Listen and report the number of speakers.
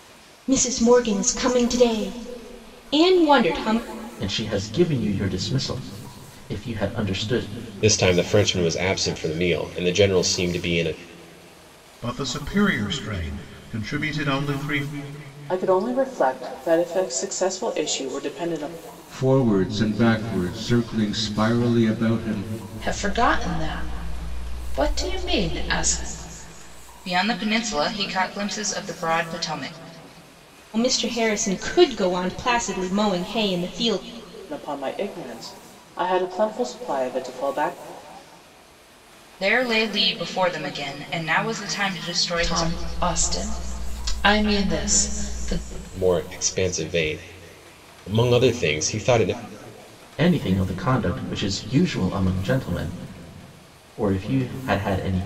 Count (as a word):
eight